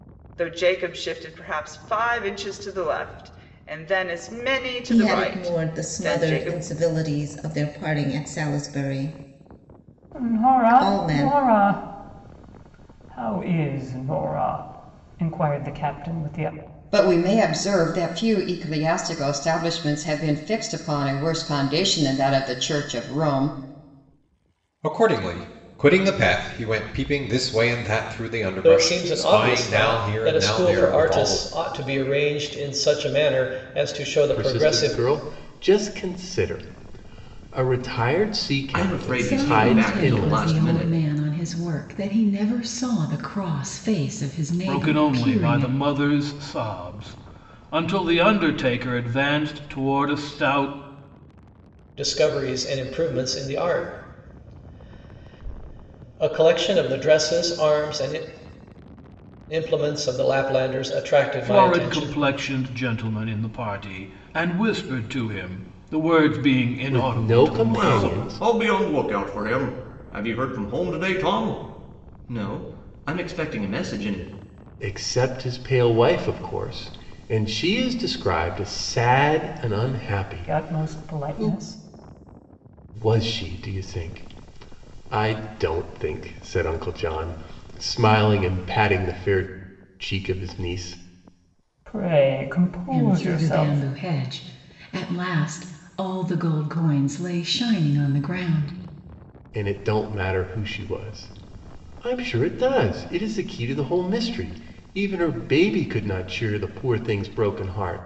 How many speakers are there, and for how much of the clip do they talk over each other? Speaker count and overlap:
ten, about 14%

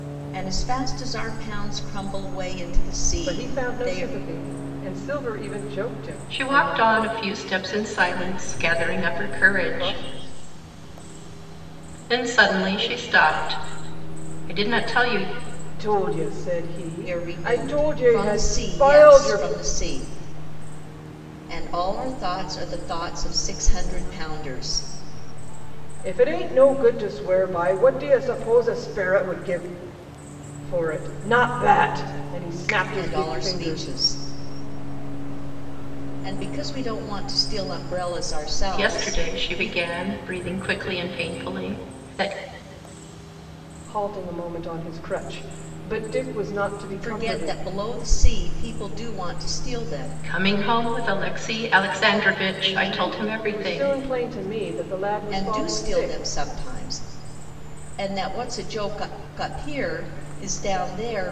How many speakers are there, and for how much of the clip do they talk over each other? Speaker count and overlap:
four, about 38%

